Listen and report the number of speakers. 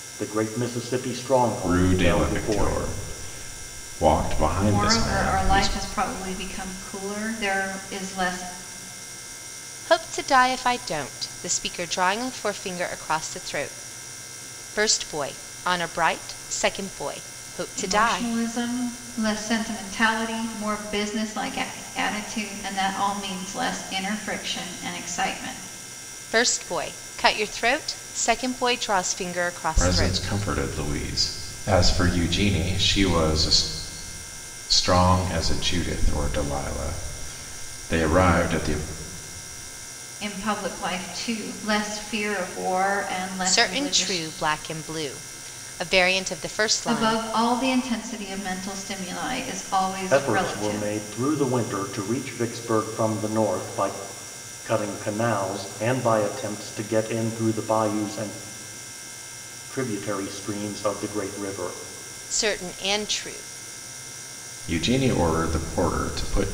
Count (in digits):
4